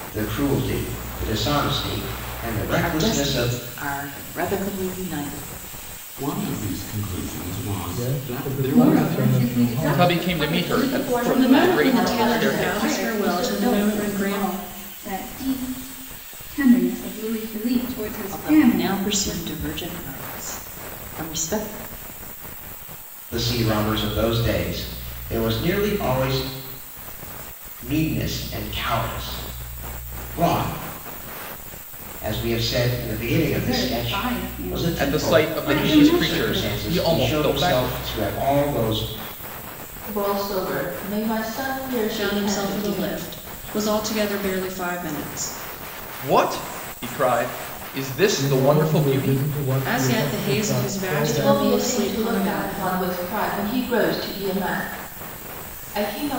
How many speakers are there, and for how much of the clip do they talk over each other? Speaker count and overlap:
8, about 33%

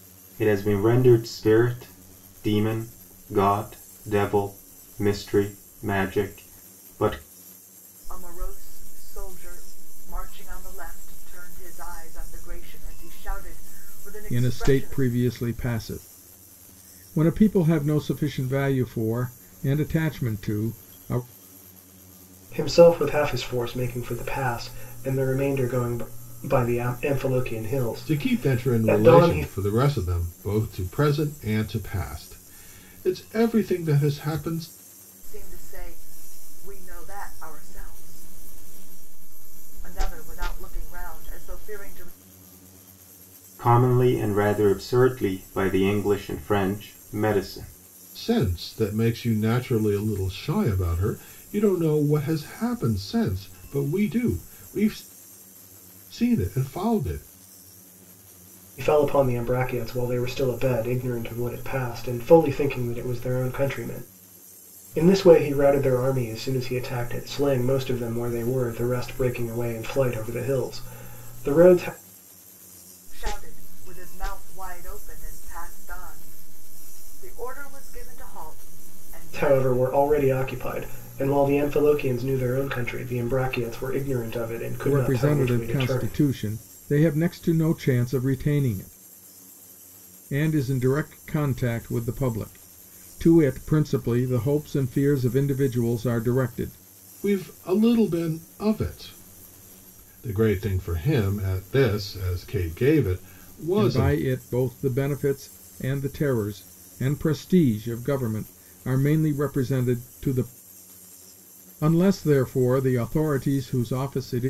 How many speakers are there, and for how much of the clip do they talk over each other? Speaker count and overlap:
5, about 4%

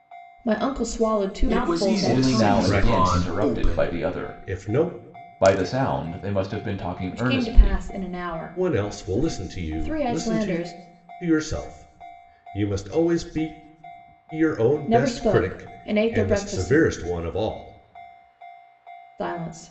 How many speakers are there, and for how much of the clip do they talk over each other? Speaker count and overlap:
4, about 37%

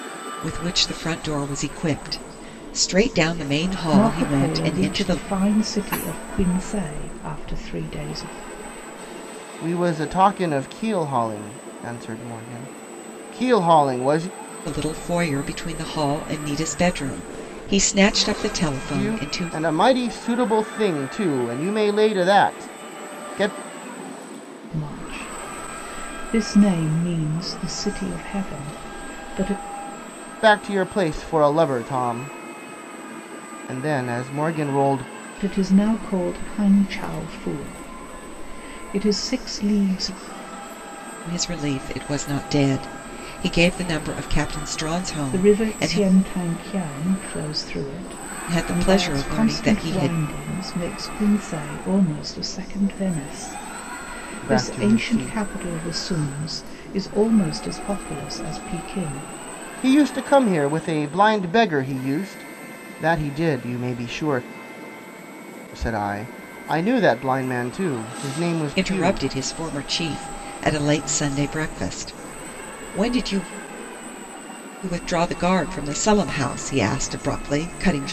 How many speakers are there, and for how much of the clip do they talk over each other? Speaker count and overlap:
3, about 8%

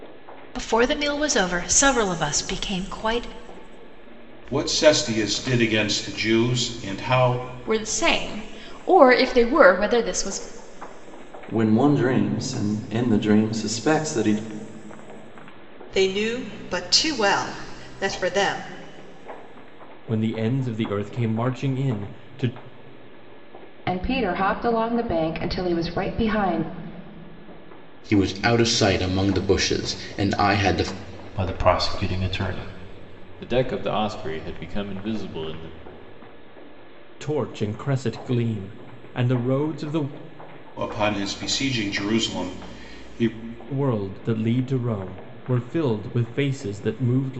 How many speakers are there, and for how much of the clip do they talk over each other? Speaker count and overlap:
10, no overlap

